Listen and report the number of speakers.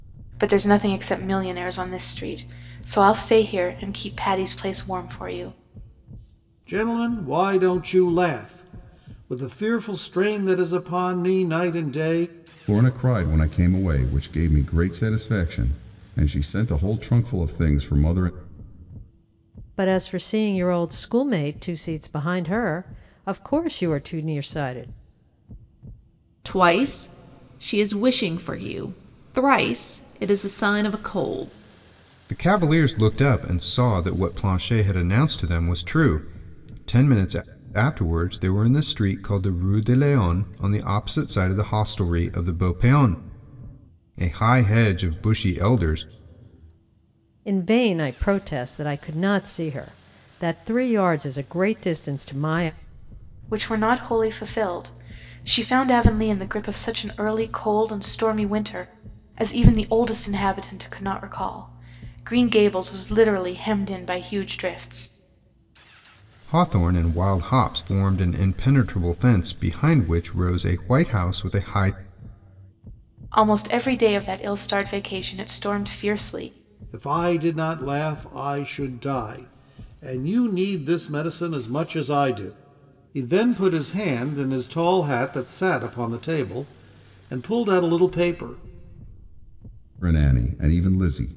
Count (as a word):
six